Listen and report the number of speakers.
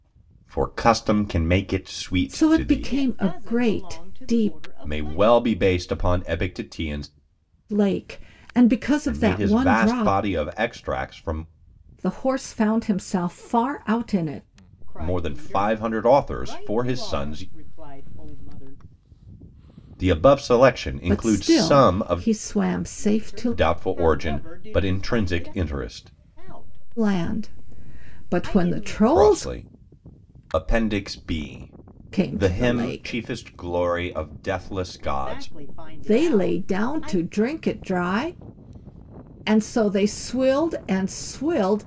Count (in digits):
3